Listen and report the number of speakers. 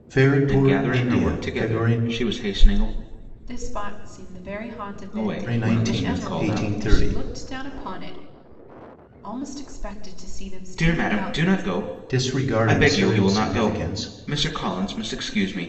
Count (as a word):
three